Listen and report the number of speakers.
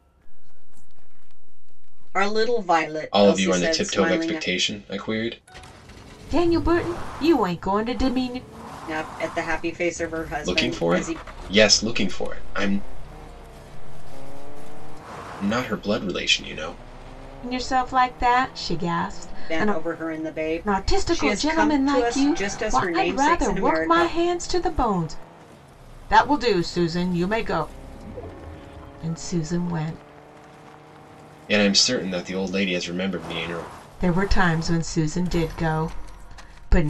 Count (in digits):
4